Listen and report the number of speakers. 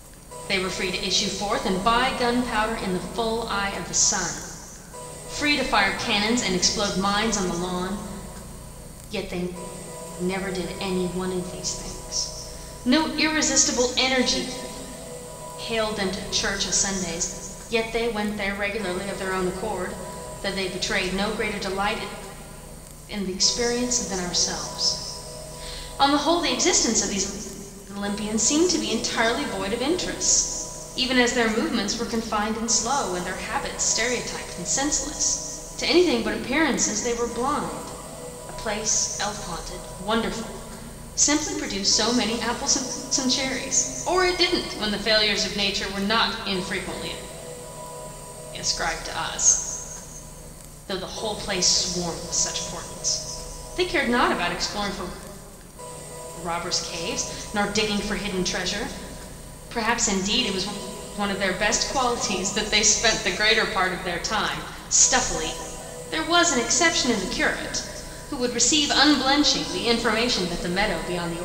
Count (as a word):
one